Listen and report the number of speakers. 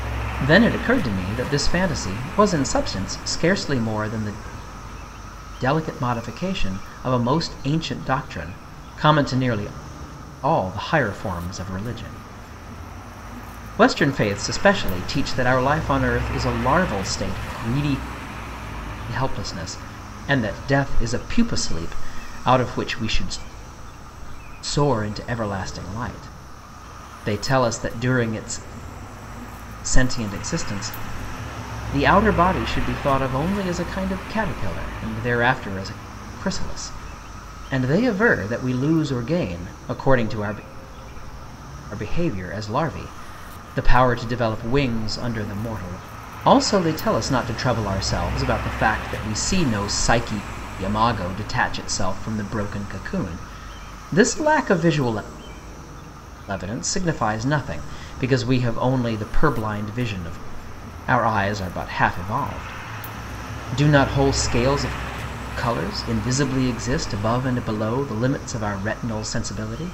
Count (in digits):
1